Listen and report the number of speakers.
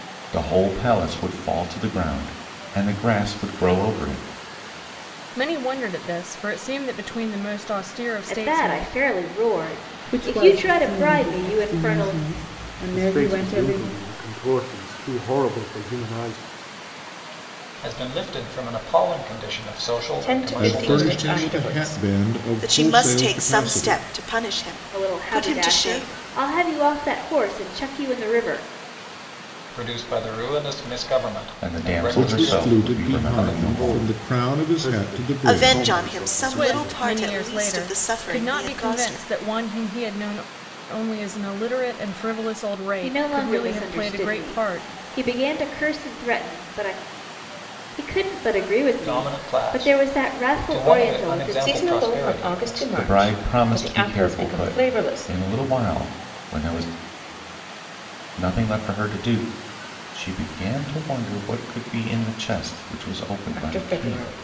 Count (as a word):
nine